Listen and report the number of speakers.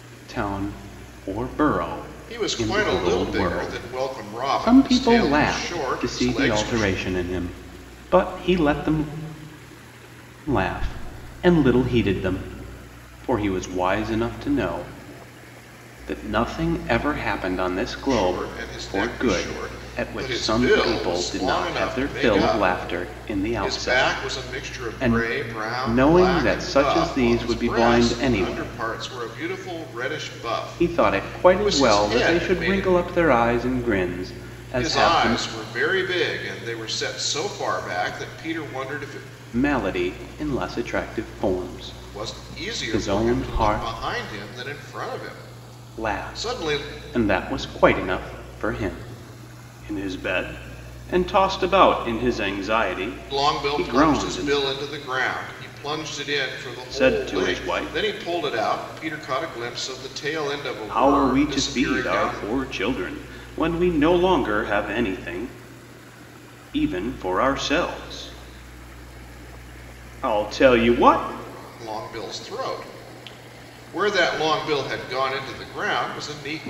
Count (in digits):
2